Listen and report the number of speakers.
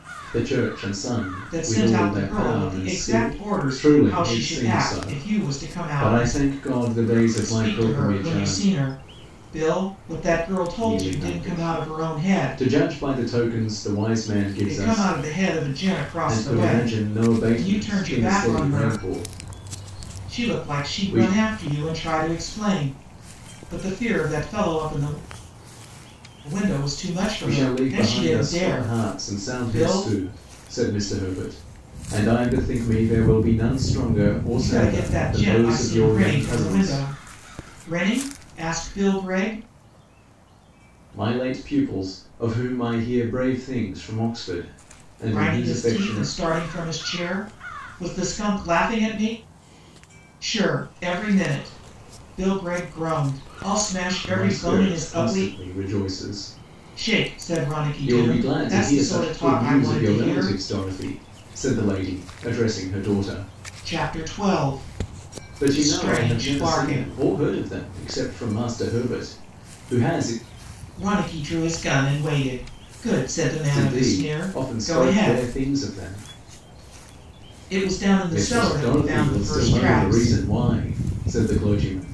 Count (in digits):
2